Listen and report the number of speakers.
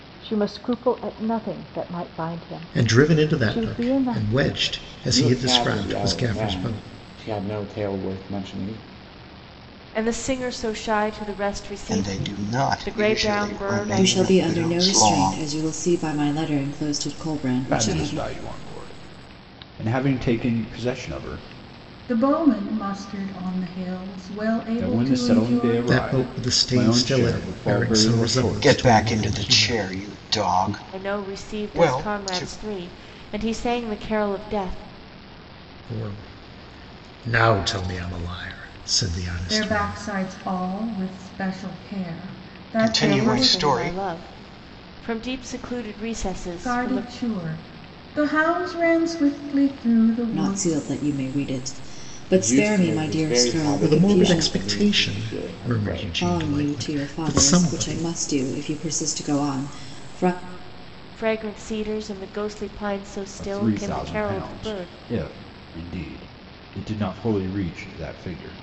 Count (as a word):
eight